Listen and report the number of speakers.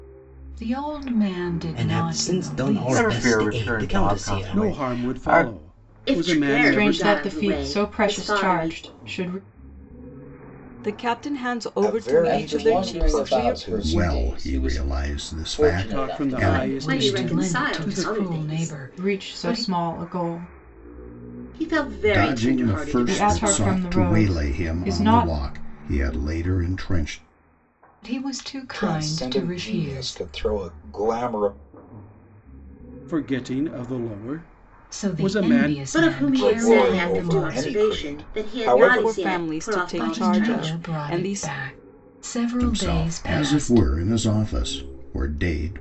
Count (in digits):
10